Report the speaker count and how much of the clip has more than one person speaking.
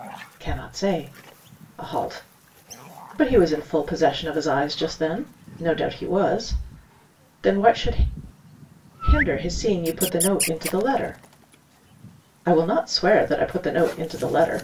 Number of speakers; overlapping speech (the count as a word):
one, no overlap